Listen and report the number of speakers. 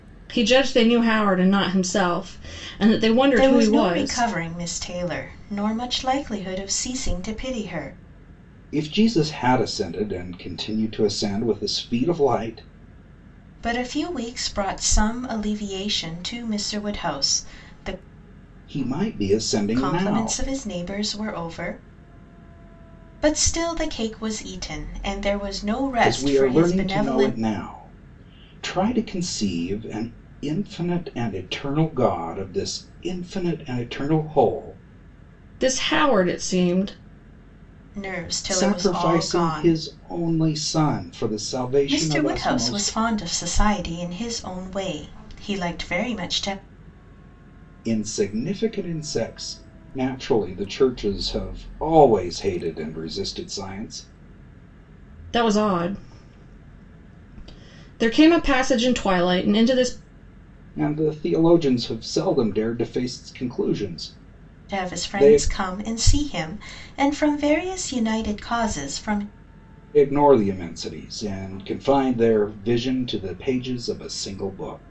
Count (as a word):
three